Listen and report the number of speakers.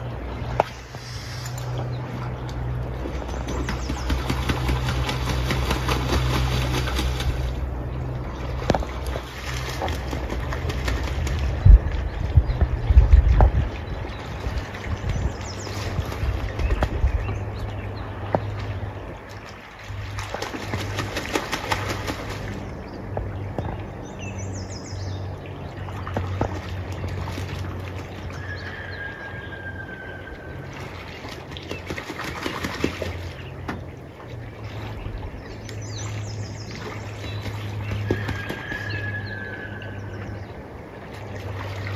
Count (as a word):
zero